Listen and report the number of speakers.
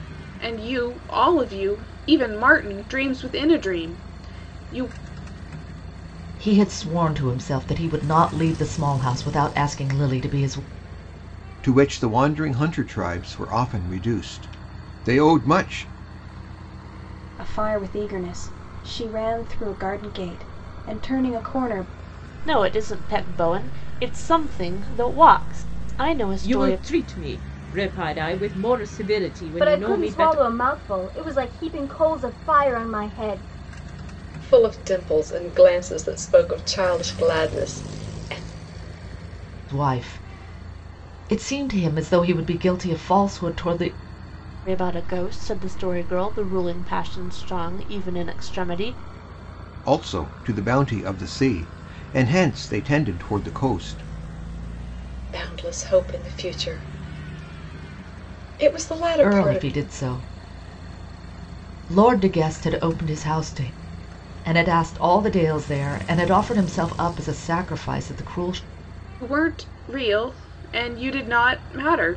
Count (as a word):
eight